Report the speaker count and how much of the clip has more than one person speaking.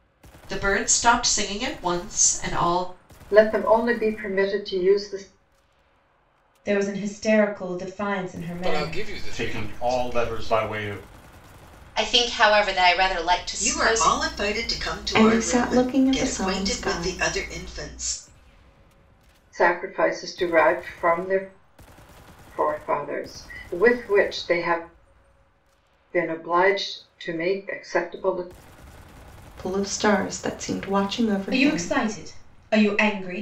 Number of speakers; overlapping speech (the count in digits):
8, about 15%